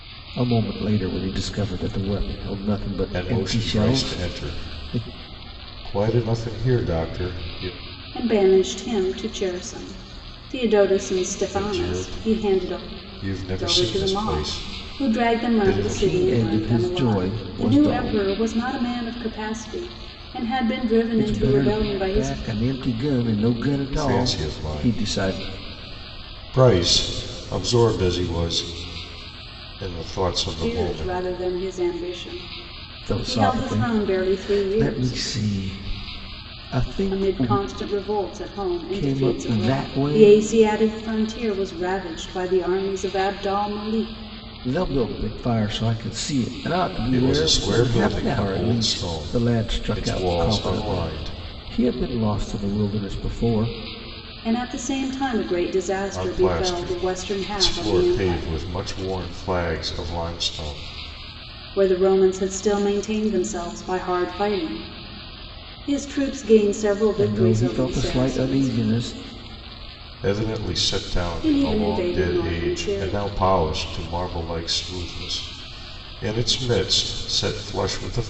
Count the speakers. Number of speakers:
3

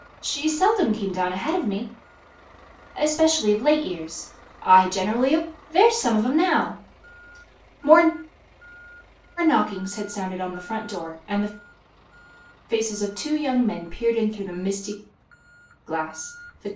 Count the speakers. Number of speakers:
1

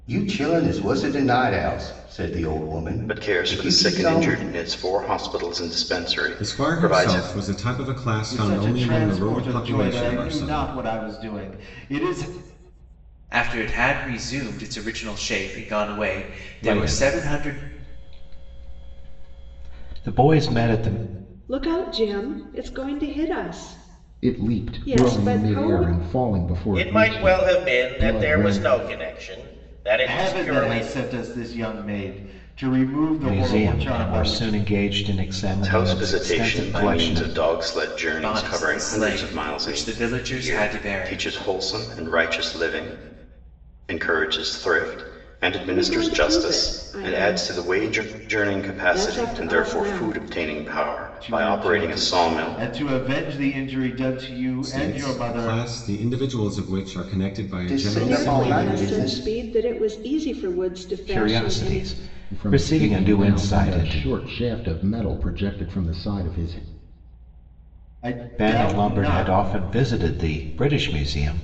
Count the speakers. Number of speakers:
9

